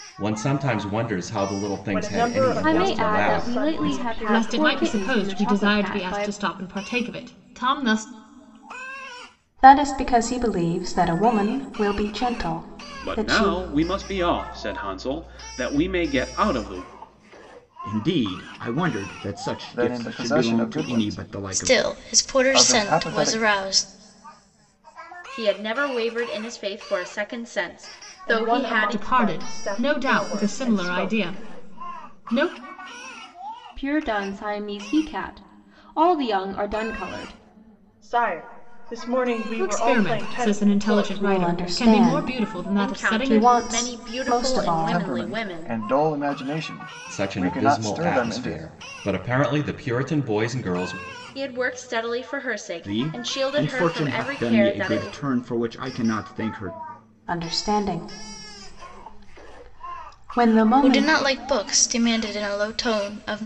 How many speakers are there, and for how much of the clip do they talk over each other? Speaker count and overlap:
10, about 37%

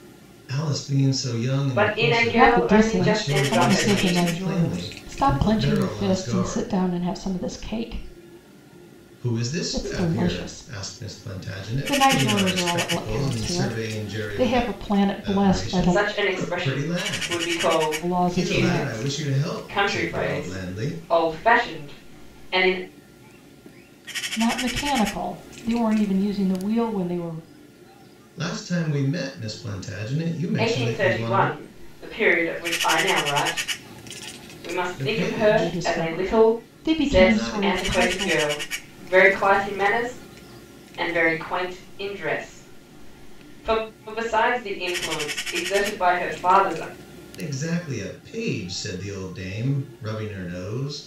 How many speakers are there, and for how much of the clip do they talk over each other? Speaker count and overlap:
3, about 37%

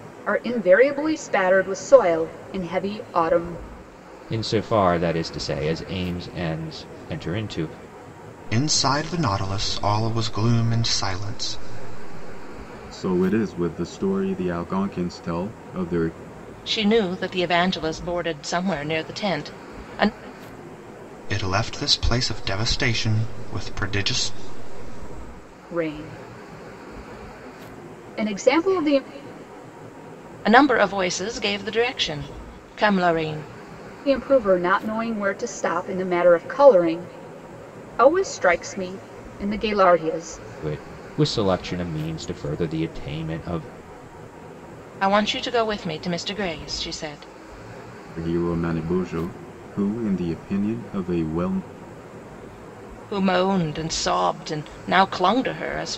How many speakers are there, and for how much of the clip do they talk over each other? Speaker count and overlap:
5, no overlap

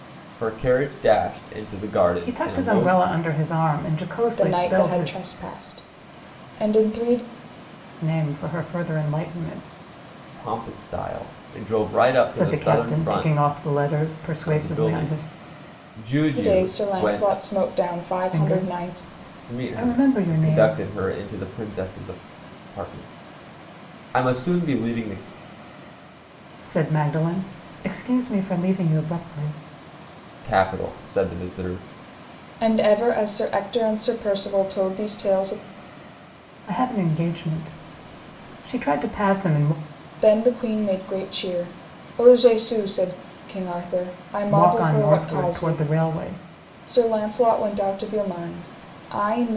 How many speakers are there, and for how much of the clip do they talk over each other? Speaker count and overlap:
3, about 17%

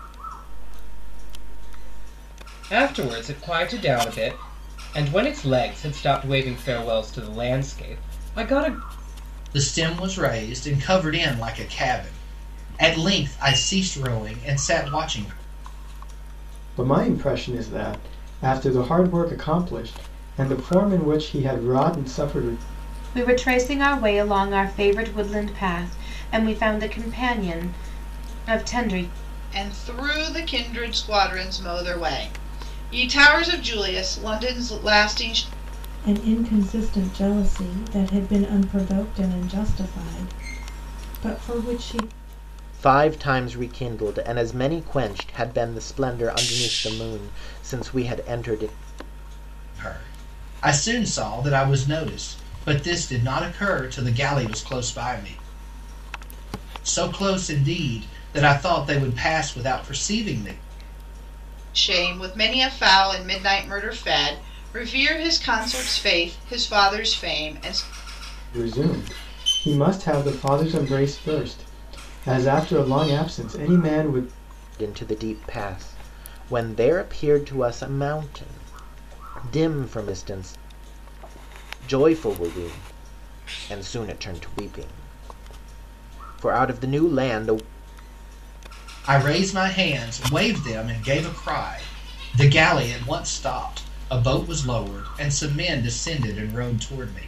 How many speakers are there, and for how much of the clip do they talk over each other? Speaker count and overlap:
8, no overlap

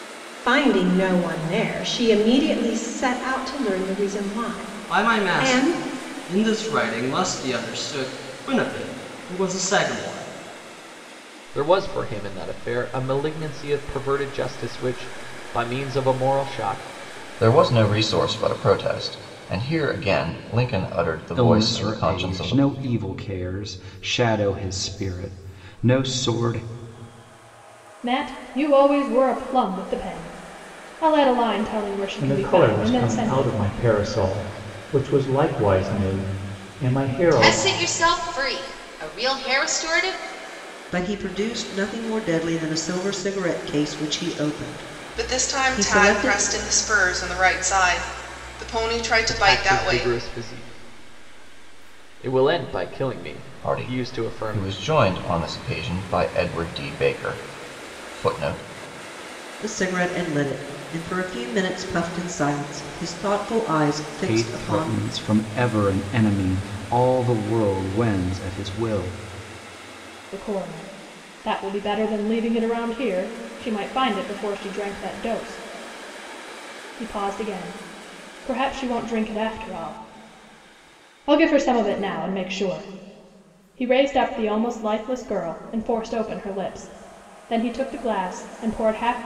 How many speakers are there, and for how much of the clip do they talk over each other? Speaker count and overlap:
10, about 9%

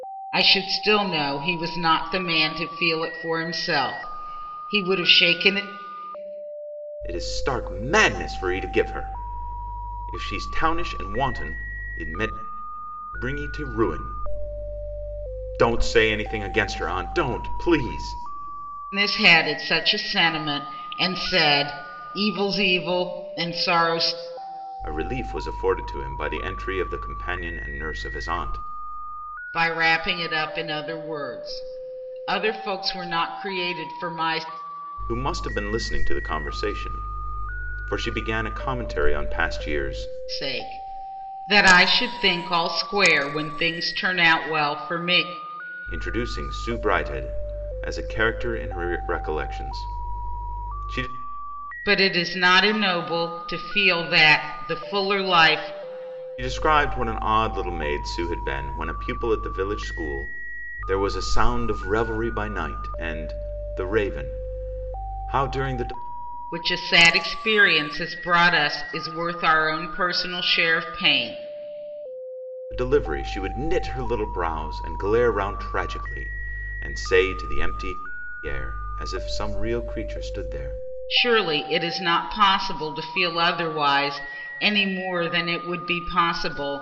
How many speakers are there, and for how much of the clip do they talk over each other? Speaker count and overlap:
2, no overlap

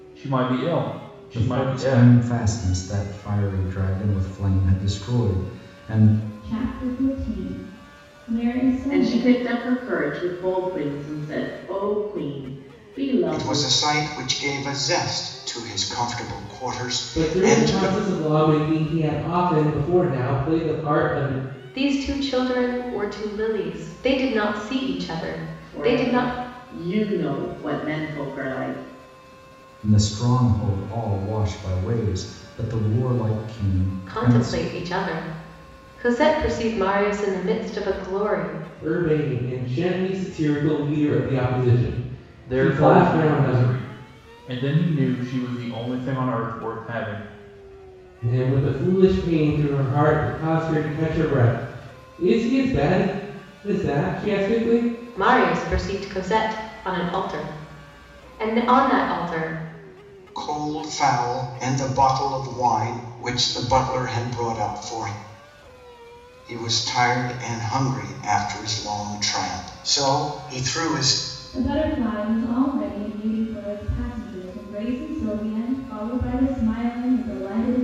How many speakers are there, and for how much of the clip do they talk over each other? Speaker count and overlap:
7, about 7%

